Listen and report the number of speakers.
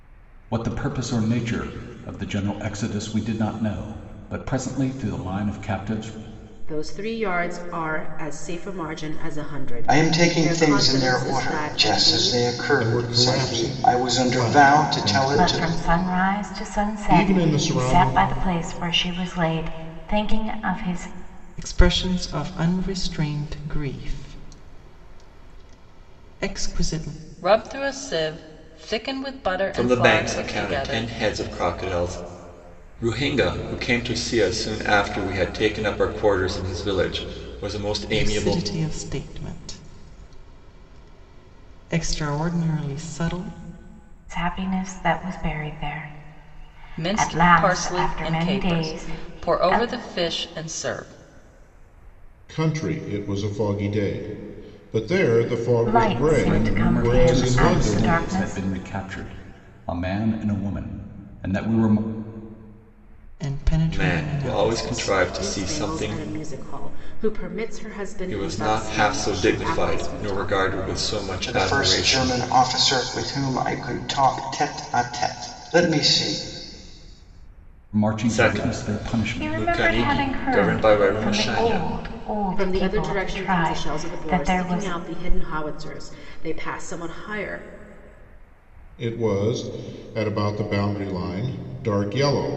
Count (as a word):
eight